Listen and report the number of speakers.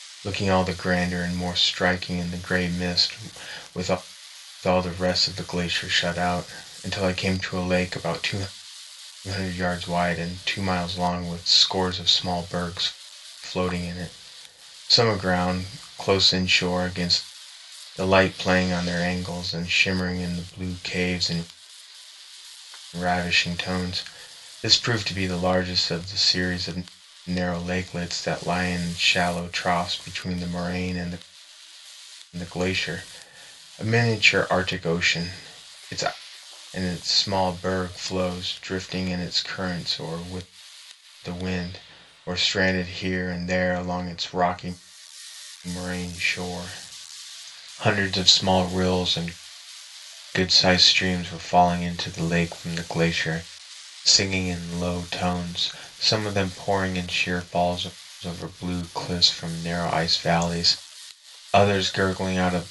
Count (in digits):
1